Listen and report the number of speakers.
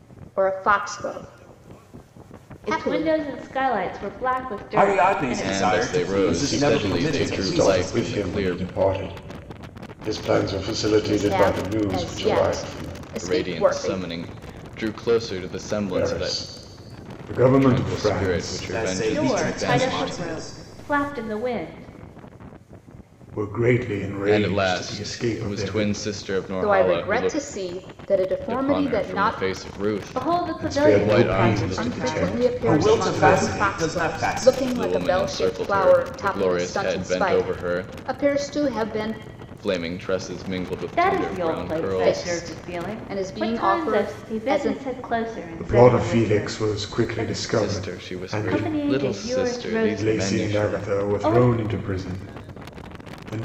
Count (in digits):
5